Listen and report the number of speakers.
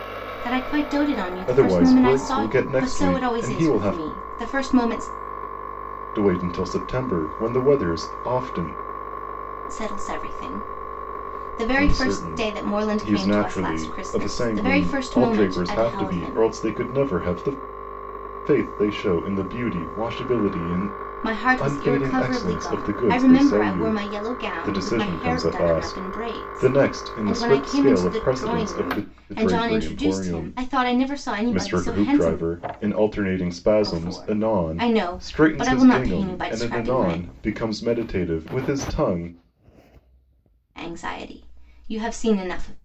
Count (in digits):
2